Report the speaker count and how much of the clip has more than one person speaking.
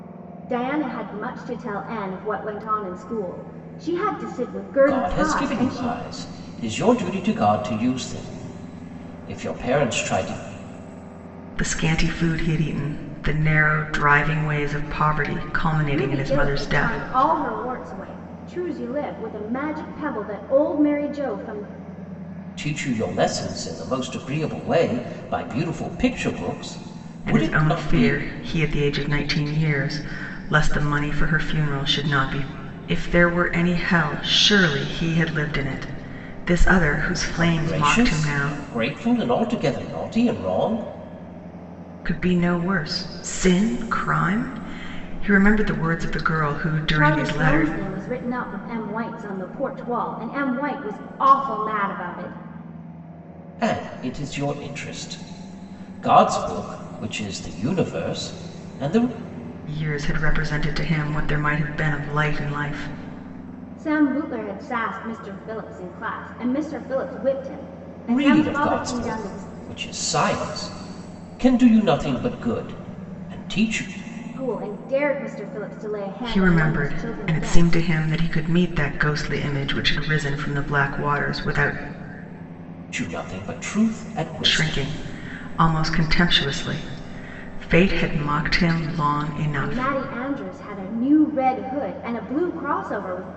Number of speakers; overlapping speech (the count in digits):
3, about 10%